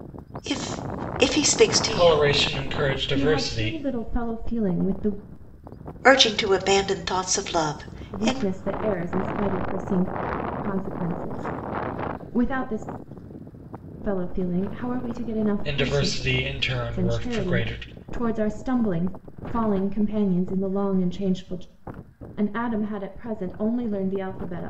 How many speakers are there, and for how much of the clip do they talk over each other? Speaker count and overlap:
3, about 13%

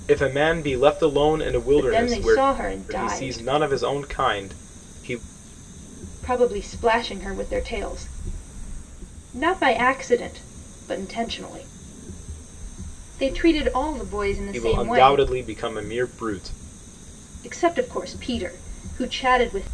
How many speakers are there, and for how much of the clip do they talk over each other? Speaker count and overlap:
2, about 10%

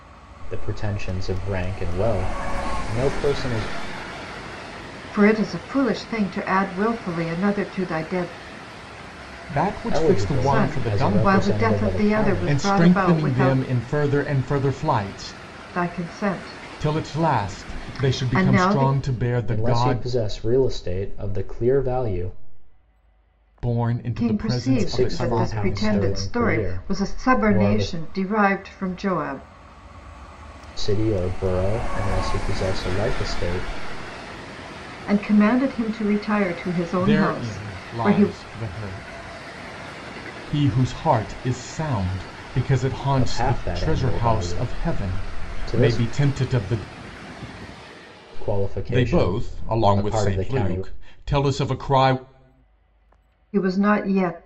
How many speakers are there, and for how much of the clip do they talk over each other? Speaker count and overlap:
3, about 31%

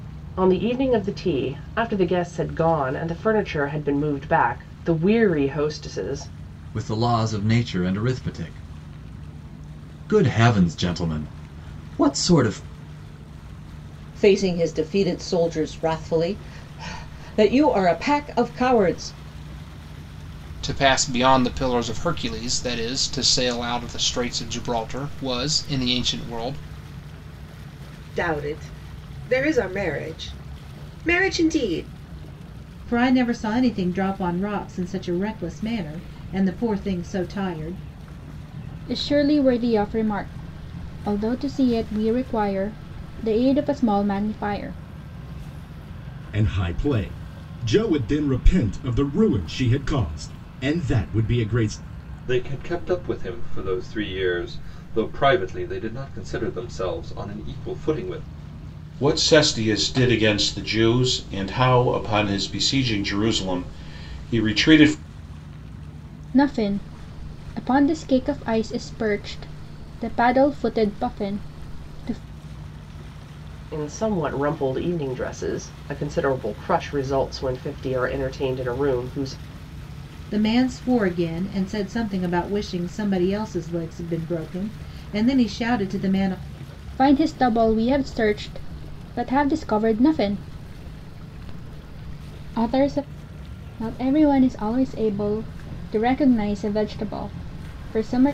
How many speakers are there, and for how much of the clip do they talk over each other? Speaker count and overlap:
10, no overlap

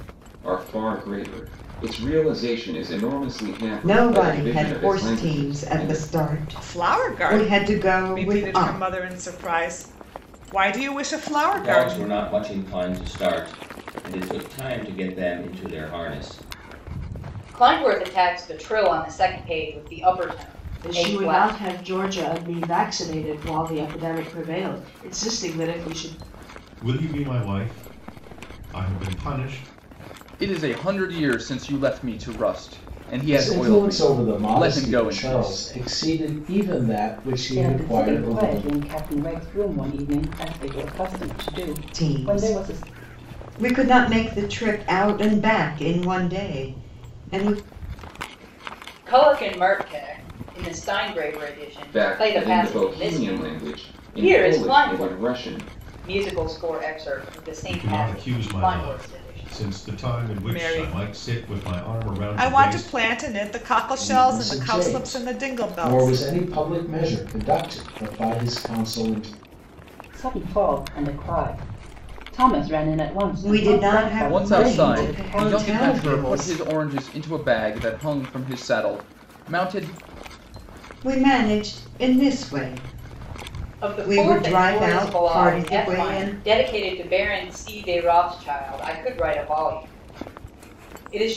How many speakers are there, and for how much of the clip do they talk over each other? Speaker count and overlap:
10, about 29%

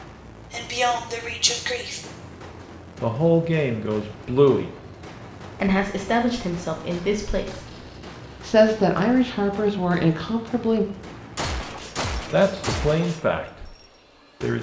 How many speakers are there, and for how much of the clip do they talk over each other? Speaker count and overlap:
4, no overlap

